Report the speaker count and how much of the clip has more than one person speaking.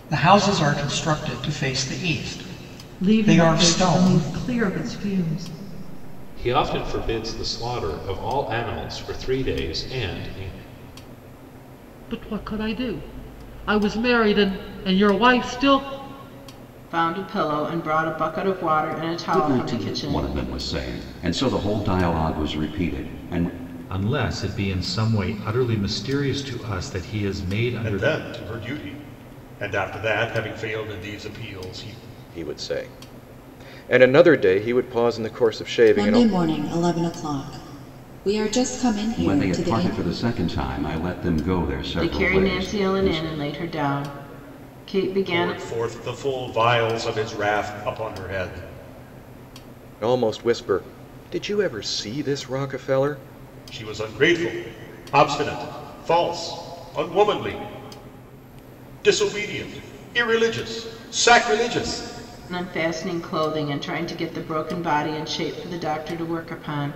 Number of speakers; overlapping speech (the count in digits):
10, about 8%